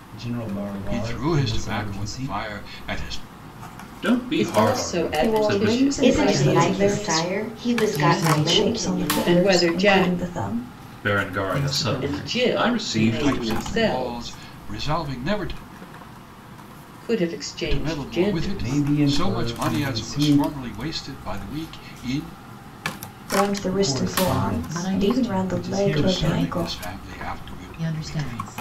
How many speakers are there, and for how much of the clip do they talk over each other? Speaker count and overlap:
7, about 59%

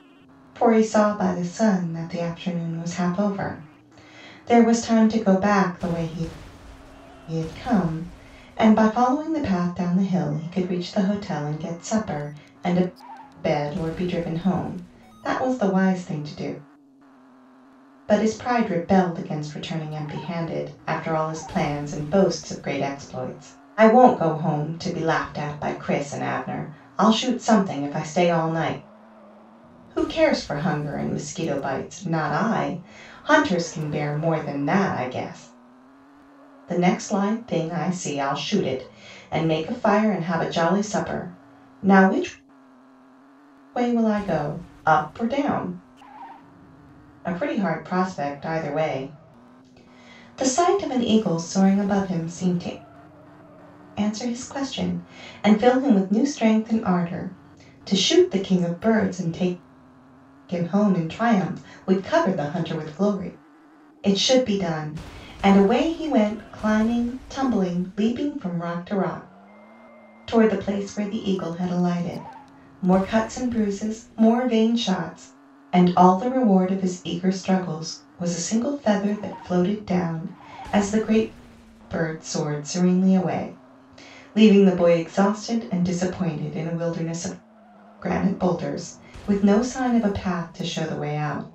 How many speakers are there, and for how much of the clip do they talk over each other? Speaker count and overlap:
1, no overlap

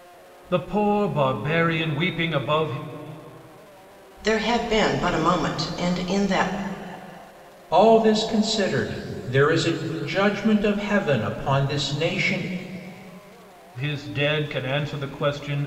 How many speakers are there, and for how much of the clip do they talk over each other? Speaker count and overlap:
3, no overlap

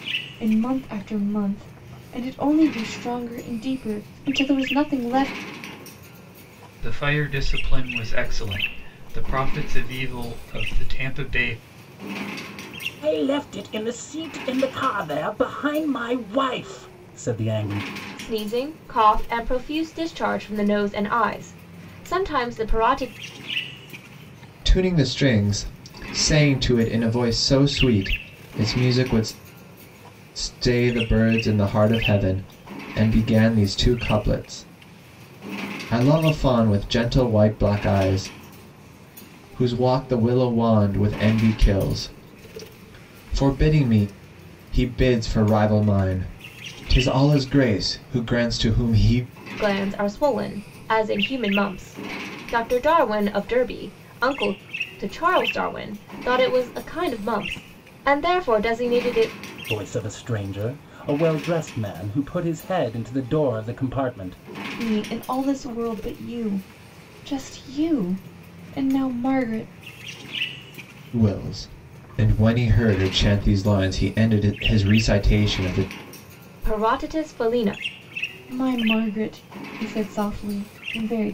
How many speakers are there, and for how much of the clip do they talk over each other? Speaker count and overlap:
5, no overlap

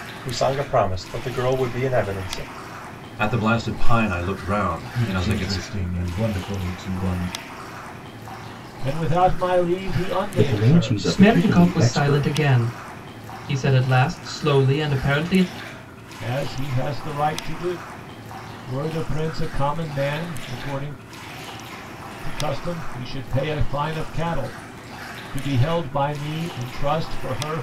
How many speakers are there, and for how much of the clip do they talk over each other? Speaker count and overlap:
6, about 10%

